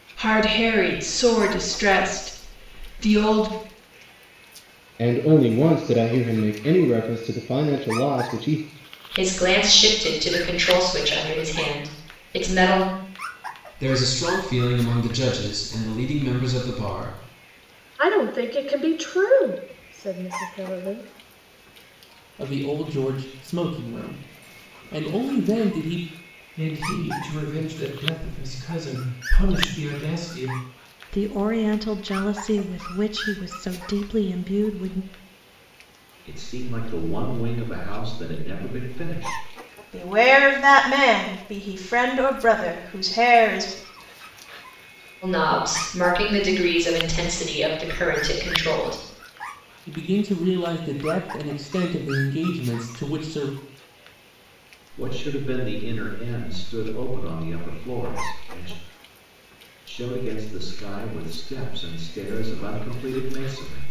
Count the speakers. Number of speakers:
10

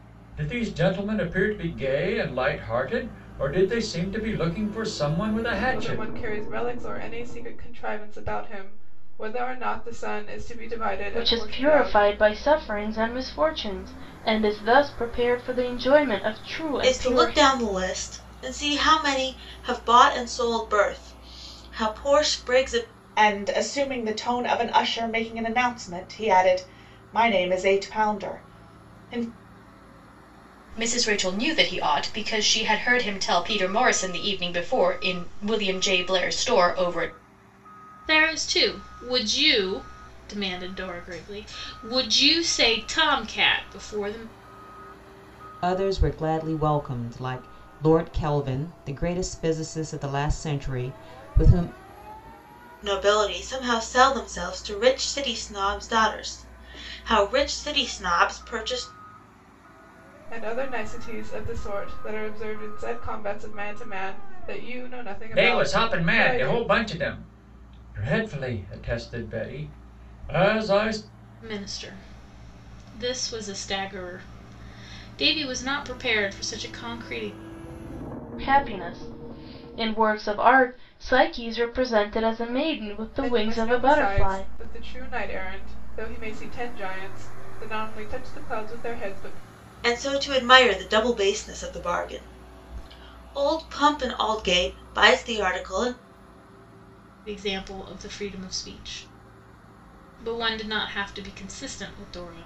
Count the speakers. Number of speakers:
8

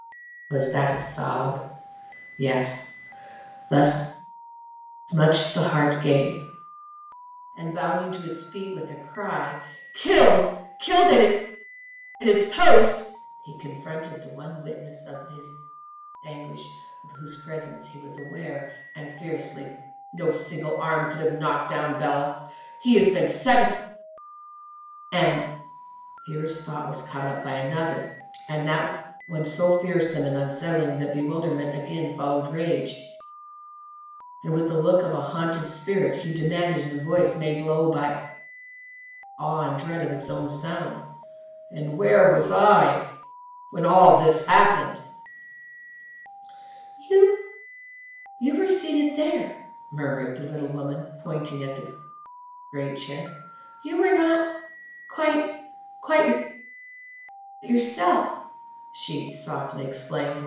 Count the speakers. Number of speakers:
1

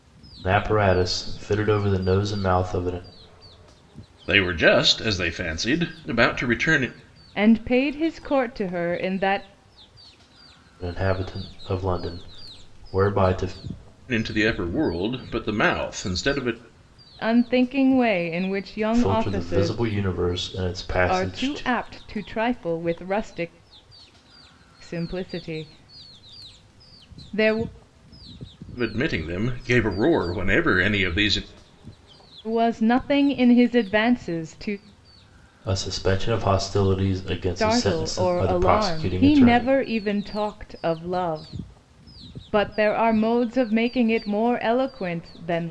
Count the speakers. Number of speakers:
3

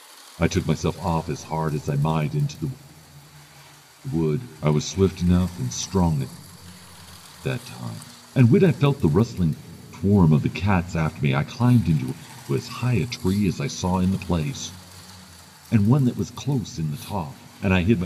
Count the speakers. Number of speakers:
1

